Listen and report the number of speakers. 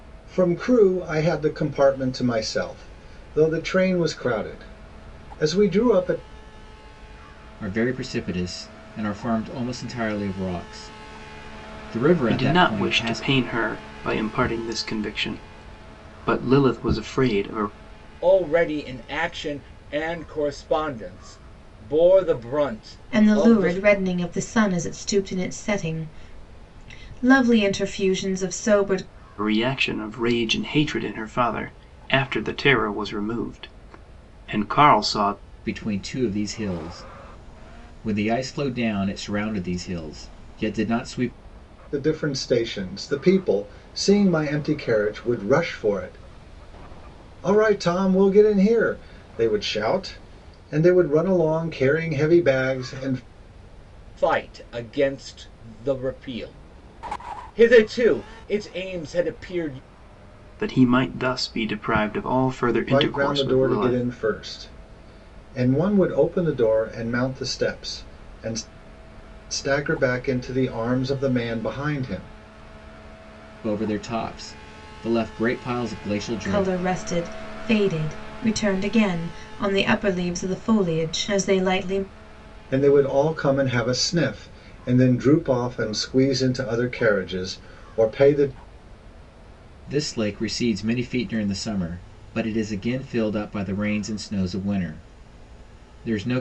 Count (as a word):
five